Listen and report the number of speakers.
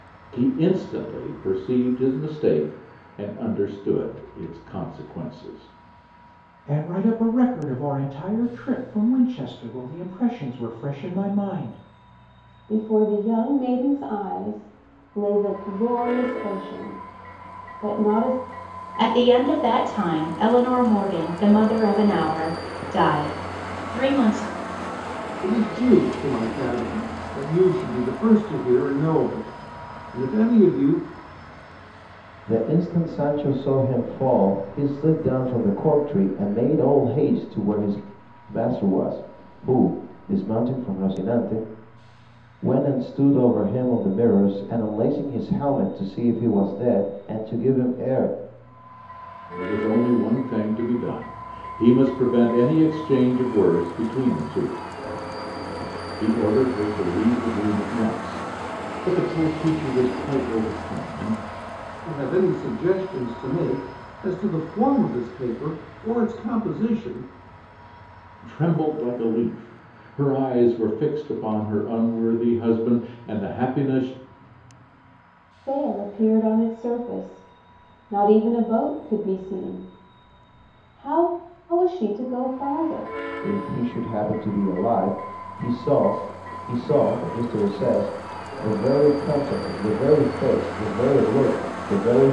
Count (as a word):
six